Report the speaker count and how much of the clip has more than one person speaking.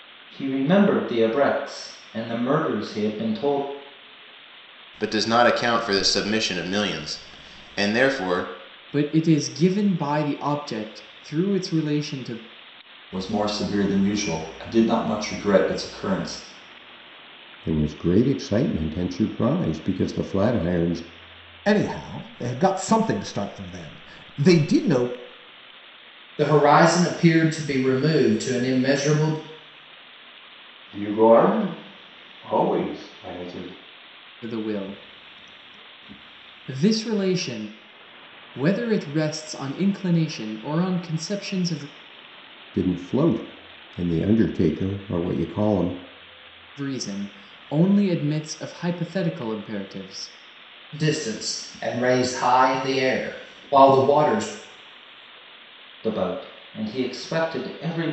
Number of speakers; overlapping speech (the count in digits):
8, no overlap